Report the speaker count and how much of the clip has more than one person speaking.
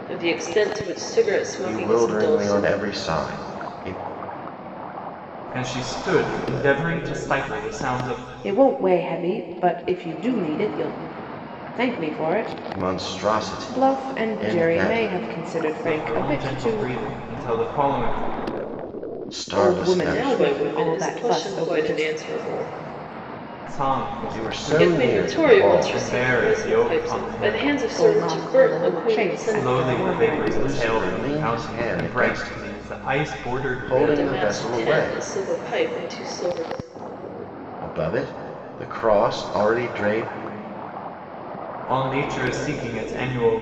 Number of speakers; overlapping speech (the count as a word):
four, about 39%